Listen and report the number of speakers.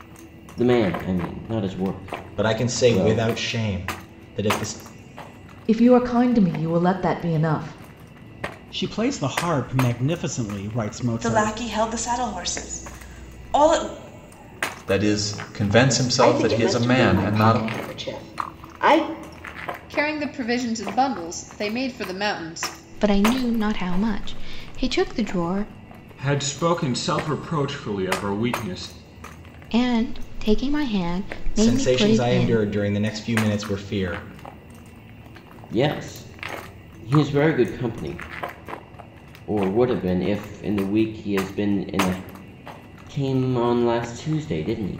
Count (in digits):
10